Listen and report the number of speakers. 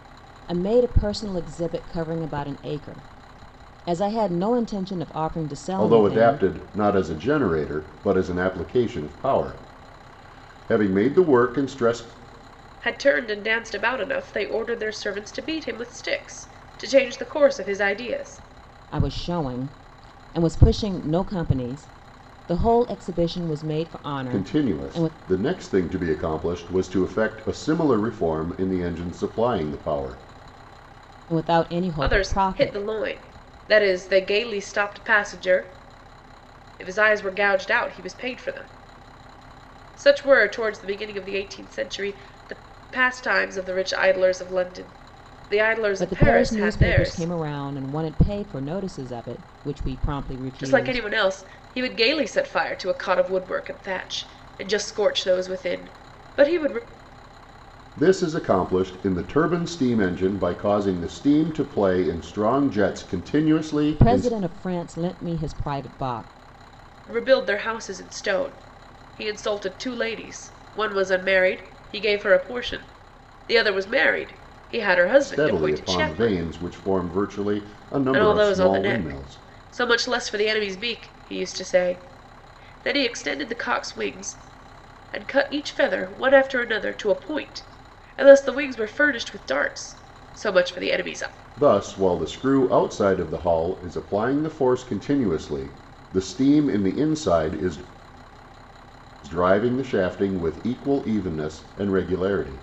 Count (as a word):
three